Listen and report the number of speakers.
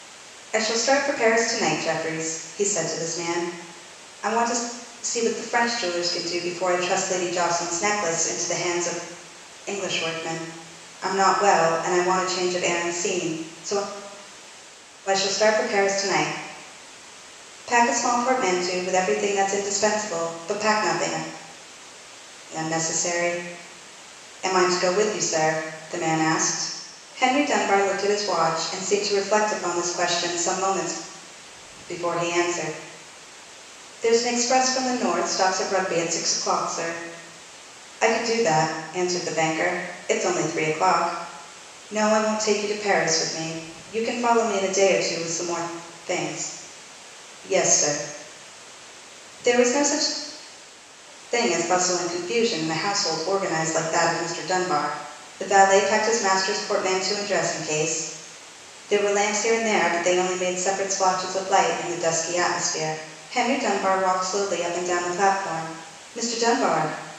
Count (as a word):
one